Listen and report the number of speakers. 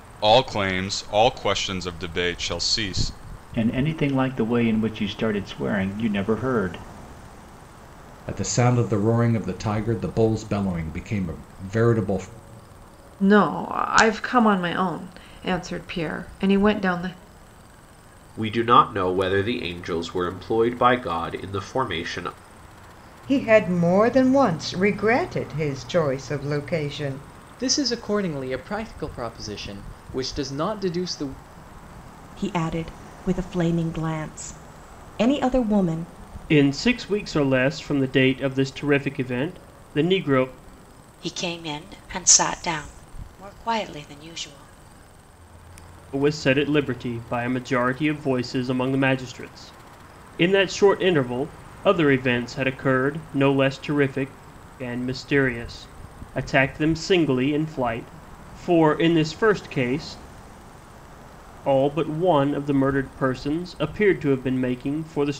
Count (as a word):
ten